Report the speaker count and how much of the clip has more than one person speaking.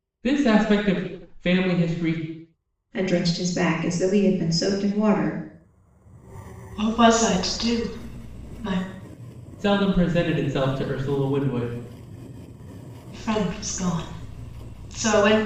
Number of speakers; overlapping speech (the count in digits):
3, no overlap